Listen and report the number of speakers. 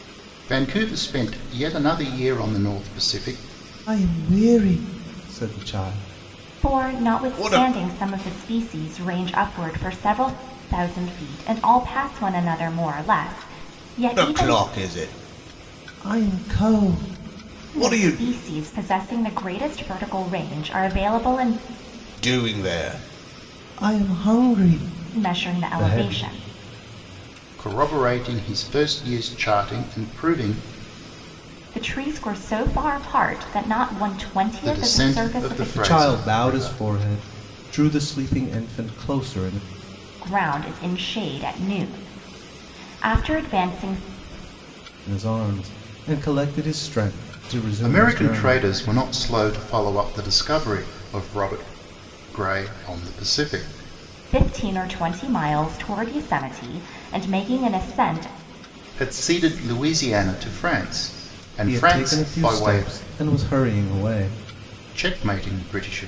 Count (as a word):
three